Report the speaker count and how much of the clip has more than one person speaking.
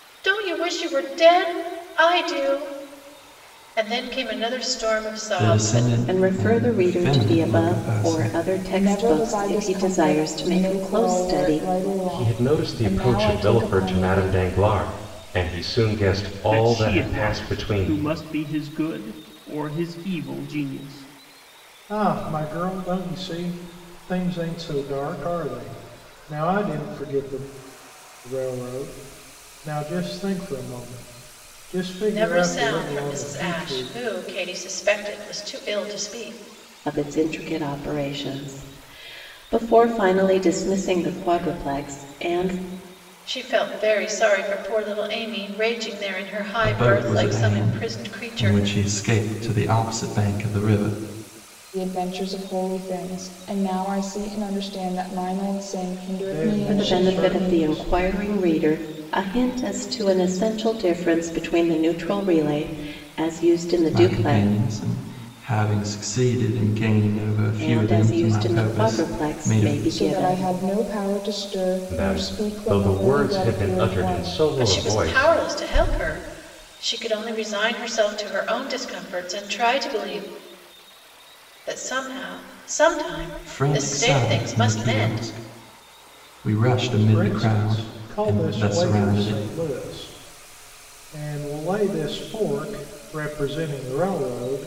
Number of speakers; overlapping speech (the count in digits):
7, about 28%